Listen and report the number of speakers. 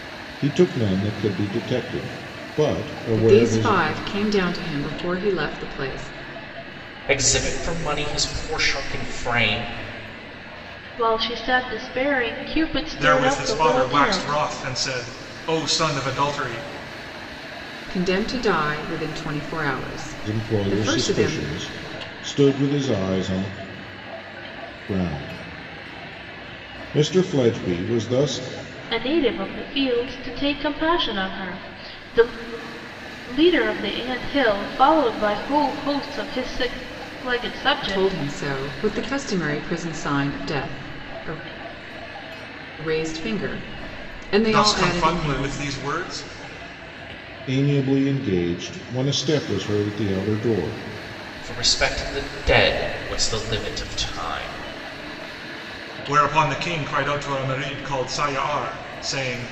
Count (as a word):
five